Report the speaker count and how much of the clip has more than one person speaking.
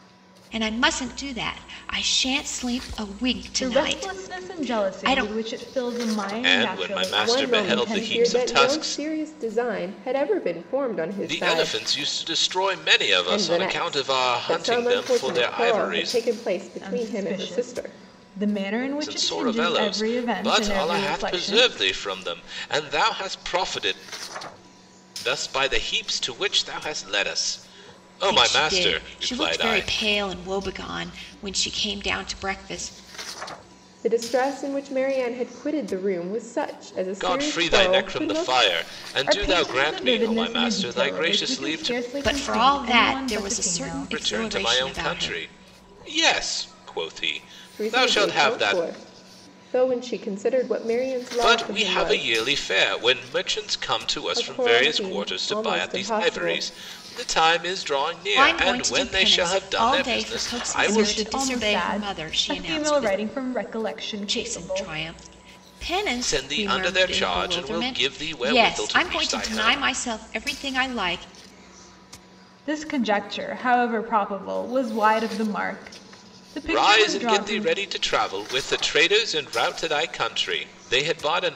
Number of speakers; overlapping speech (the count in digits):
4, about 44%